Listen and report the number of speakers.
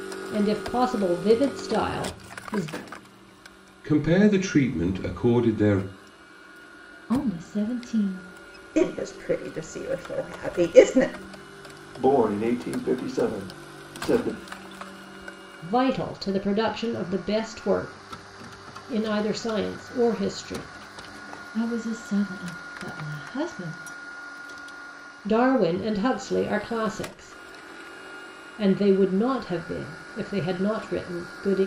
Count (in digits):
5